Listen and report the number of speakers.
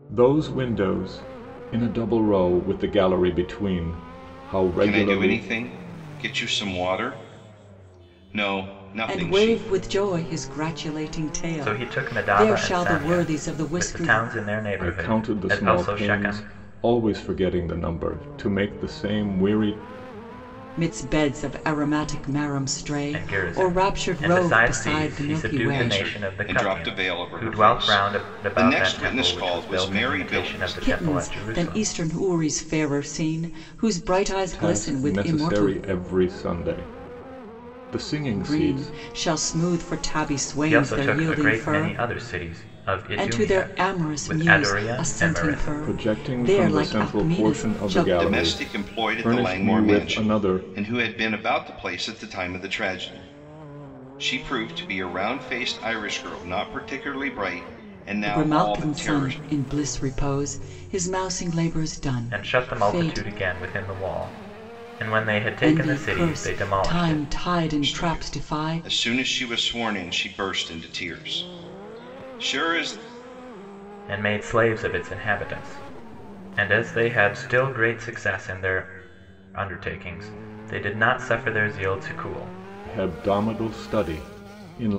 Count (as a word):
four